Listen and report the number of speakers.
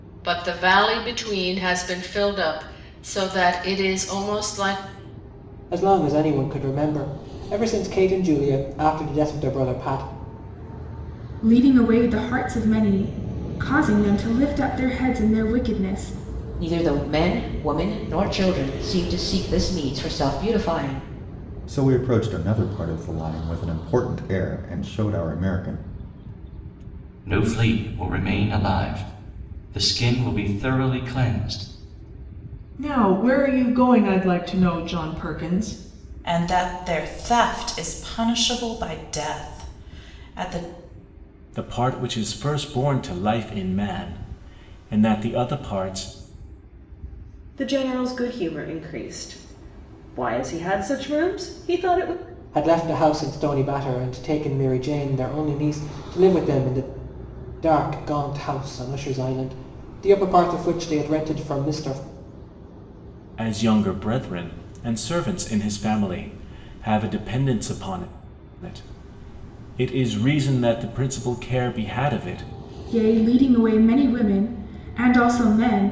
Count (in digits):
10